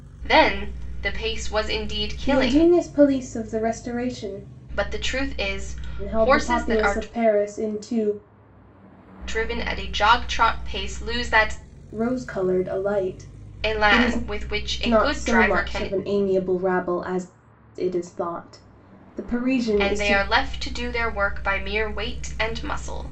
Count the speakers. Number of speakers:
2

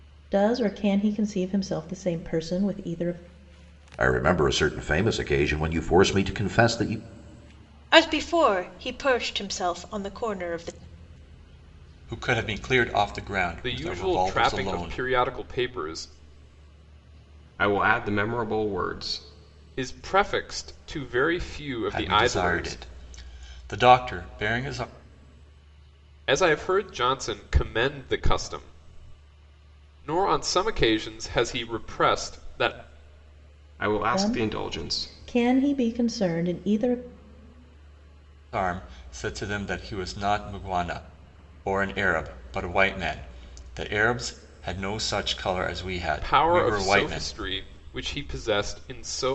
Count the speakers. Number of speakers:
6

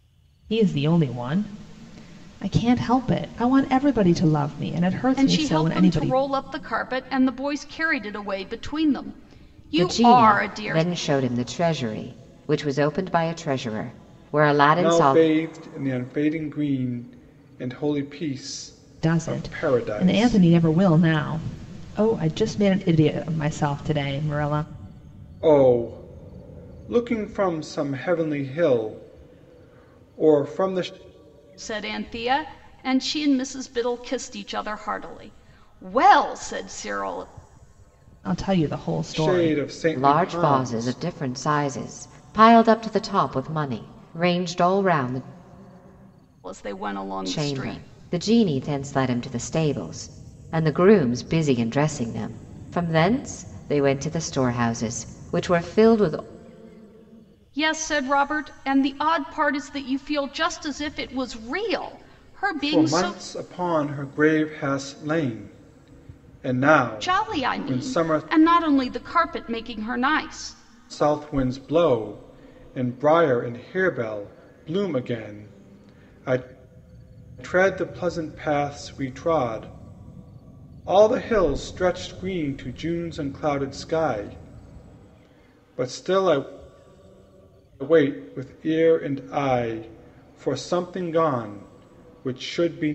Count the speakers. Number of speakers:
4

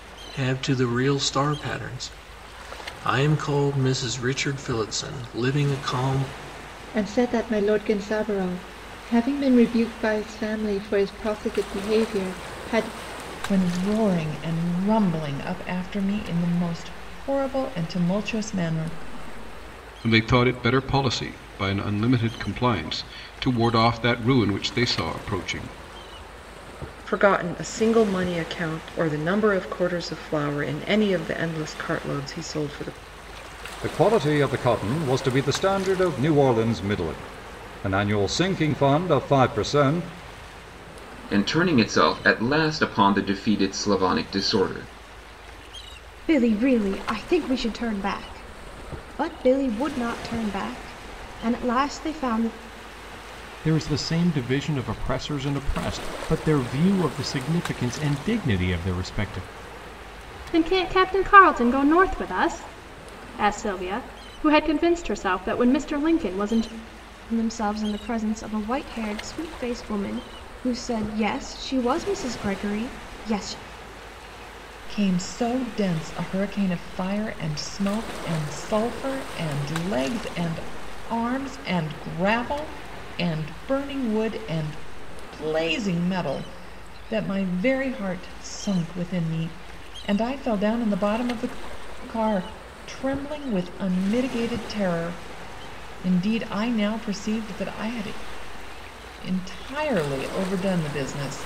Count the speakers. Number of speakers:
10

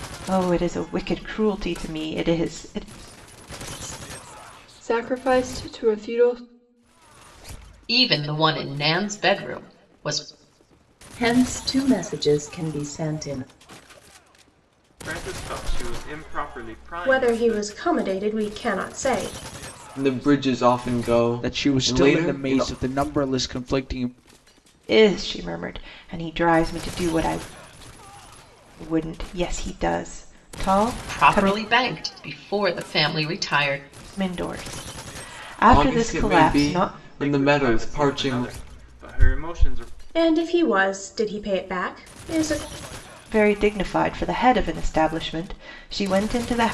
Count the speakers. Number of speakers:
8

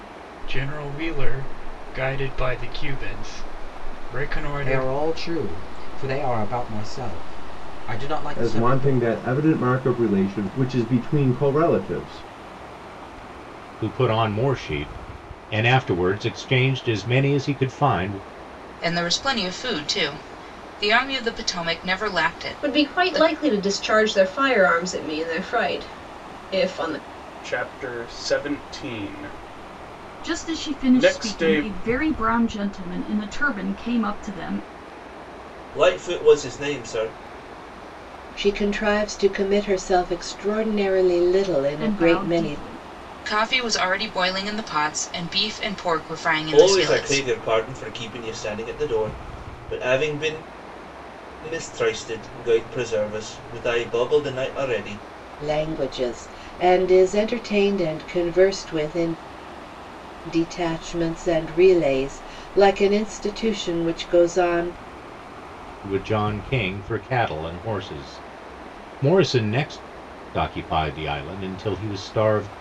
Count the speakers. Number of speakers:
10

